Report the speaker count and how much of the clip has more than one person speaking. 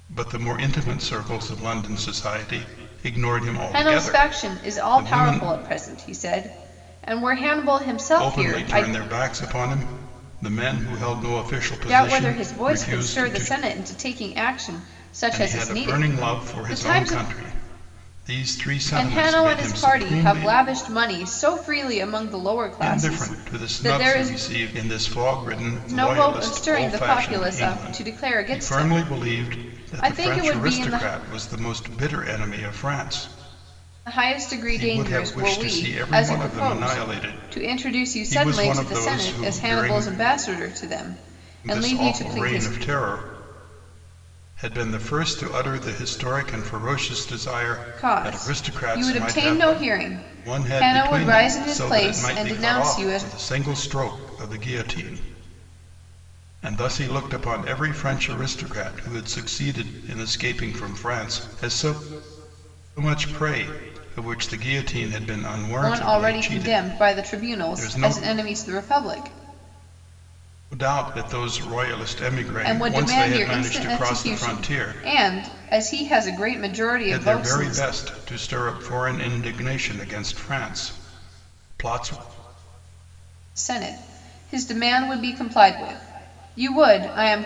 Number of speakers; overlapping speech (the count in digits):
2, about 35%